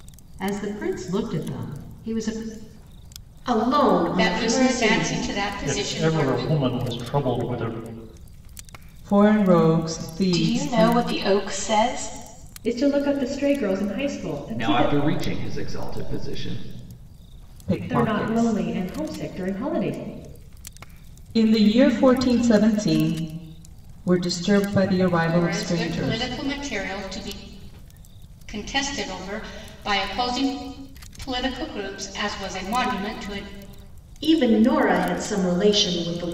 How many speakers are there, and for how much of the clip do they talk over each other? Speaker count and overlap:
eight, about 14%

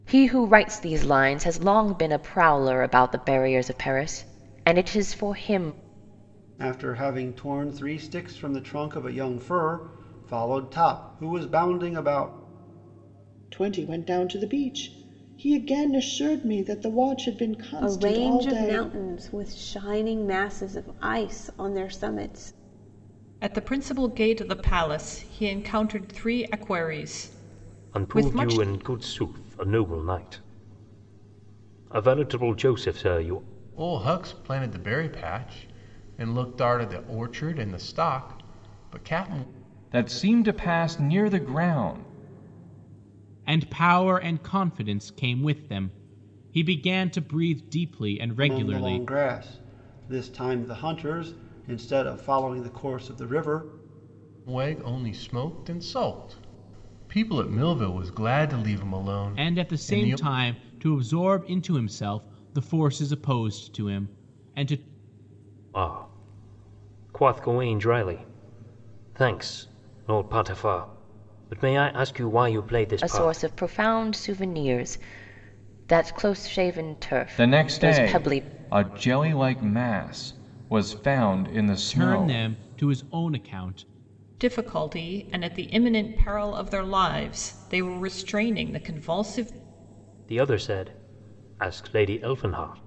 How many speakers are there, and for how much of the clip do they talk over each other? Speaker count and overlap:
nine, about 6%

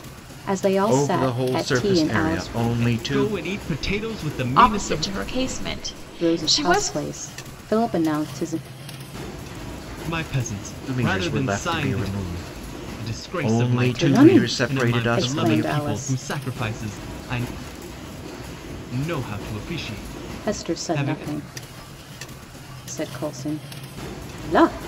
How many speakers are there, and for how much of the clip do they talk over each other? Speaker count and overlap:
four, about 34%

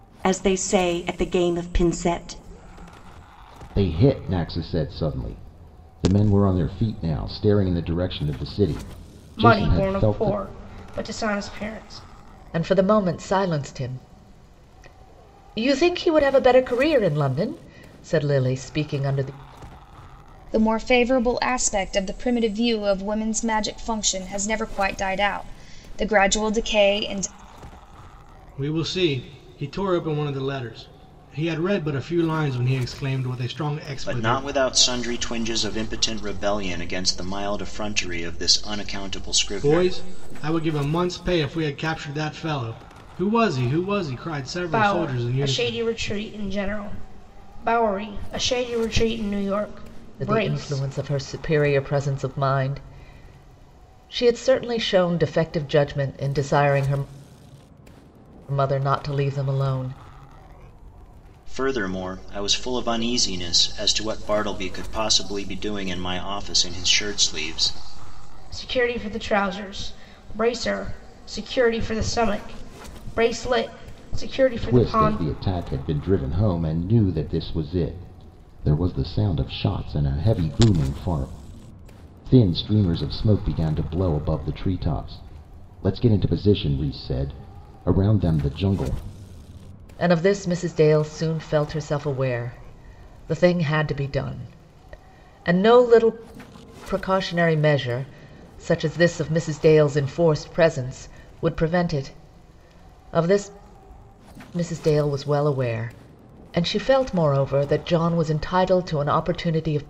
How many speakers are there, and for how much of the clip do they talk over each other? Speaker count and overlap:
seven, about 4%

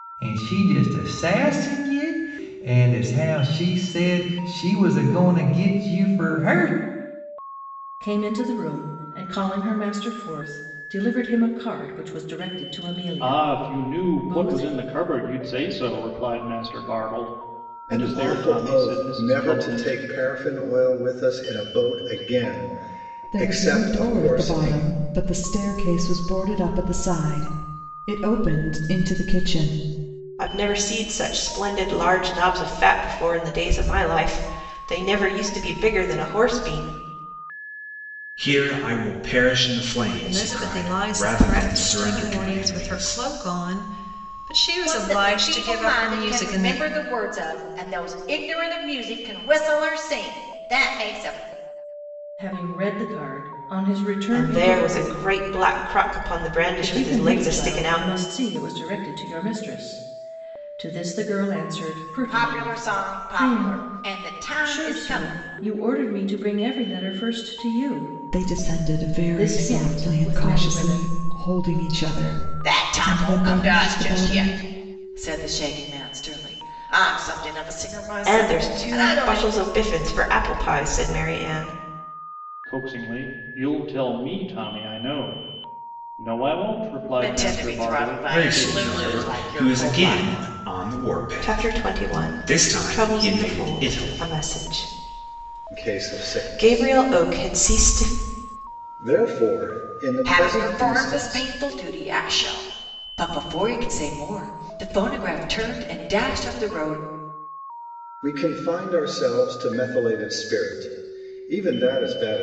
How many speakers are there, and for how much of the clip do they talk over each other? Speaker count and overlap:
nine, about 28%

